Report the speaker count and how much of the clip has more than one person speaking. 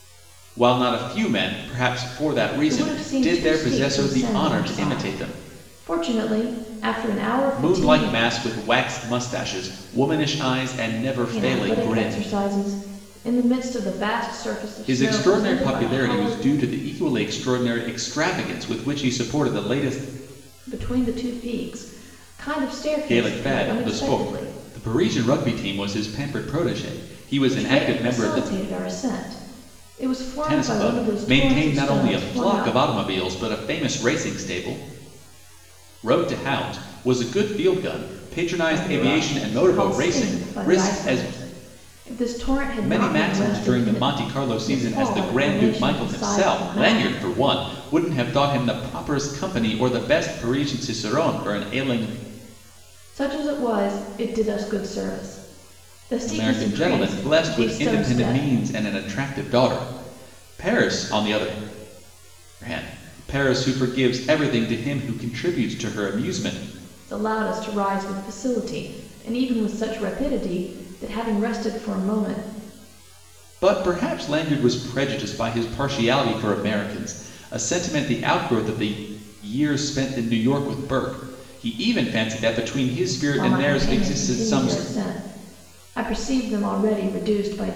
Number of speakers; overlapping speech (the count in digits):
2, about 24%